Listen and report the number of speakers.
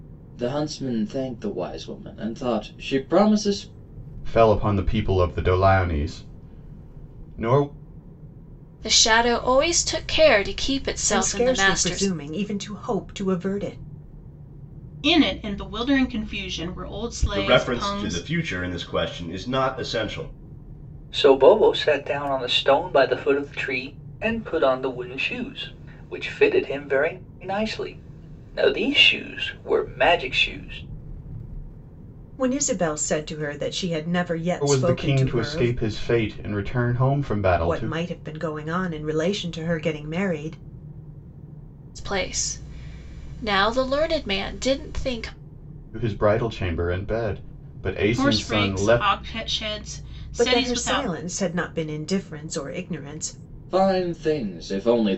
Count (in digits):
7